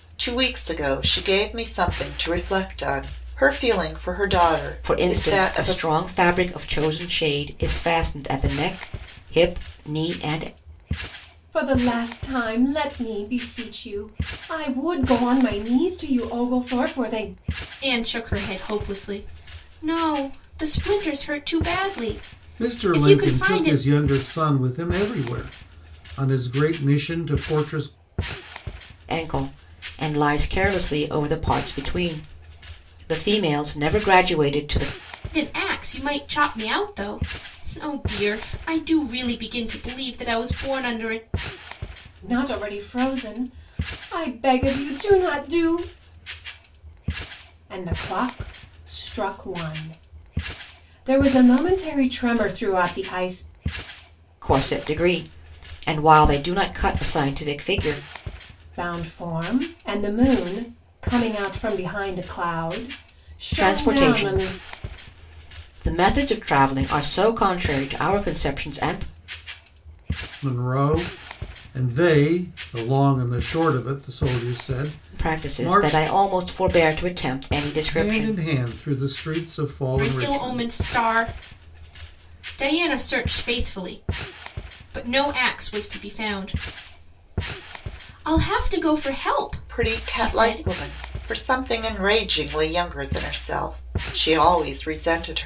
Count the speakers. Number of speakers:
five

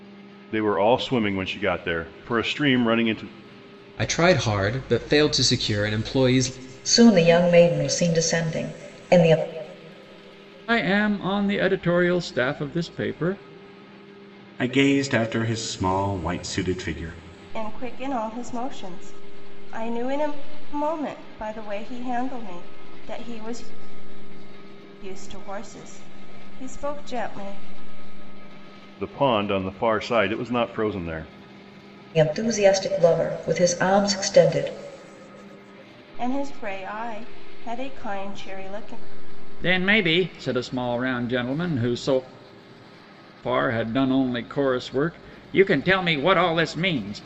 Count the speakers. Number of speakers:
six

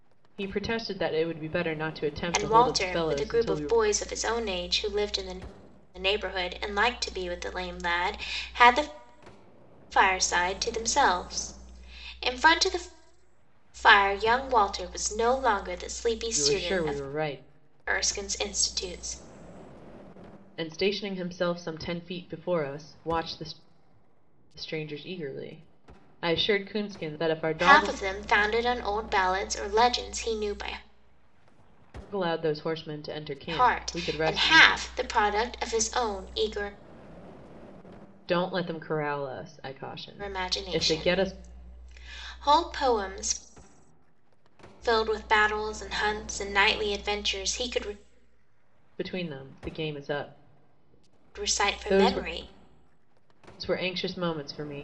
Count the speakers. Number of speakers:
two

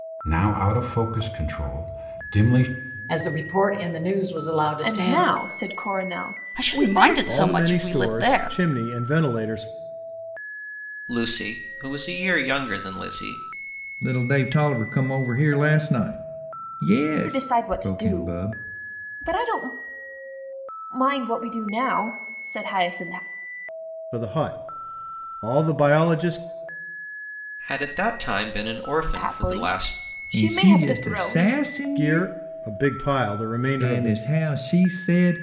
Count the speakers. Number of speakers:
seven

